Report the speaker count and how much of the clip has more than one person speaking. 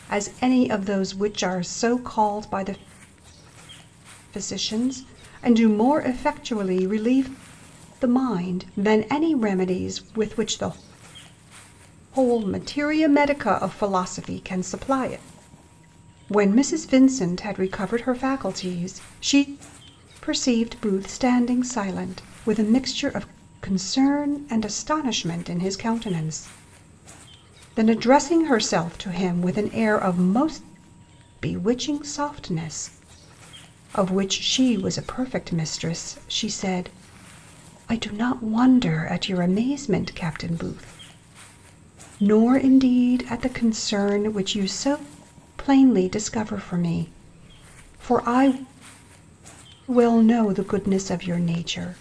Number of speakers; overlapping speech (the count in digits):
1, no overlap